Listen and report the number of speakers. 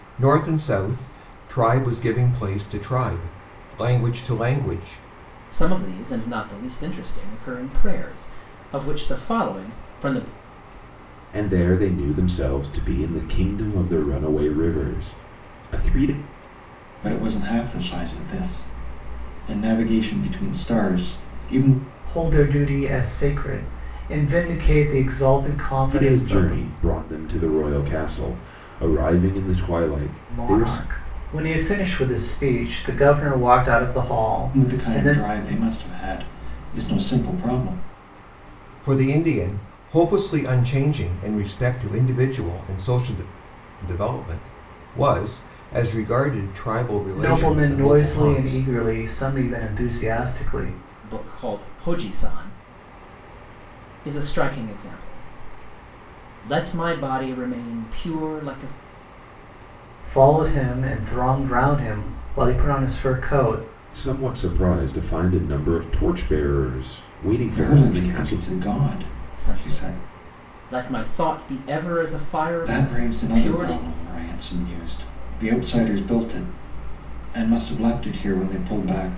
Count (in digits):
5